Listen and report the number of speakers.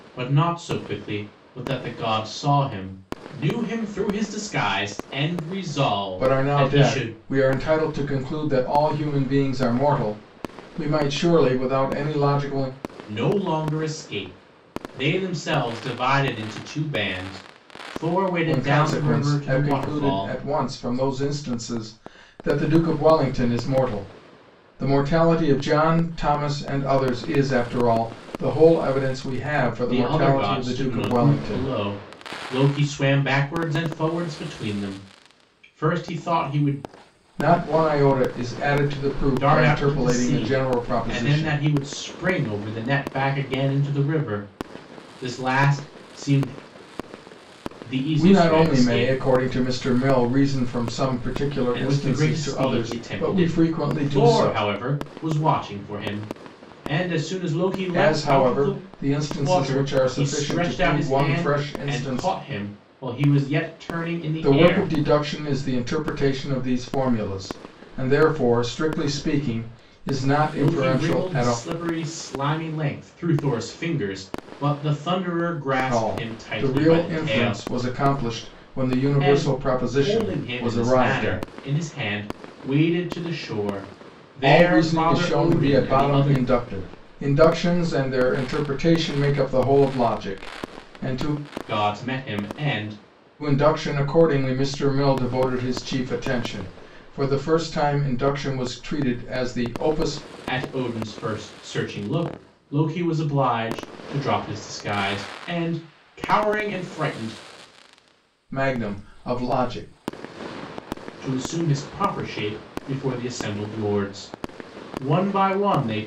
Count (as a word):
two